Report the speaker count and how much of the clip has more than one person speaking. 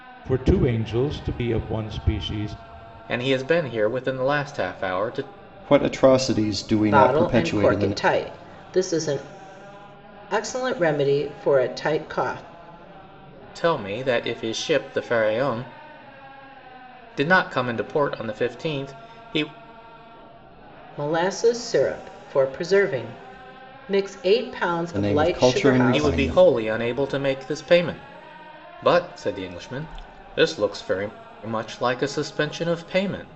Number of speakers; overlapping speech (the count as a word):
four, about 8%